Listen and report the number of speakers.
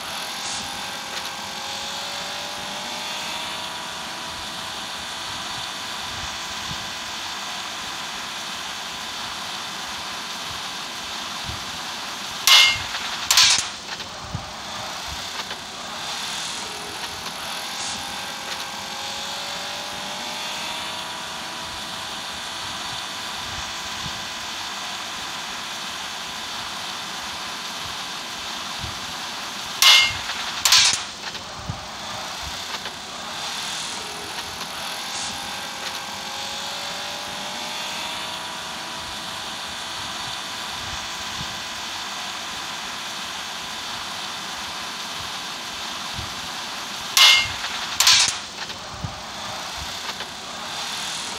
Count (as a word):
zero